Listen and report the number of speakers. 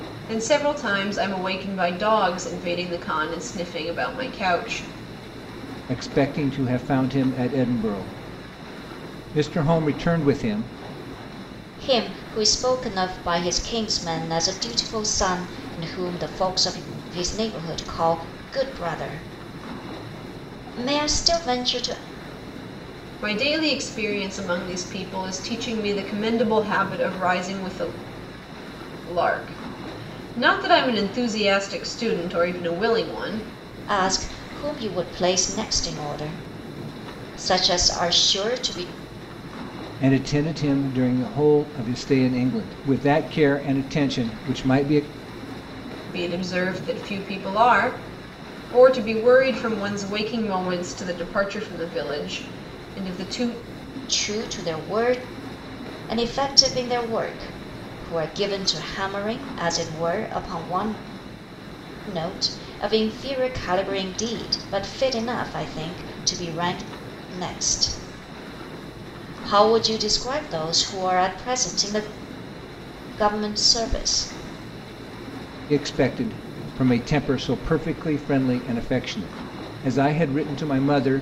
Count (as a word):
three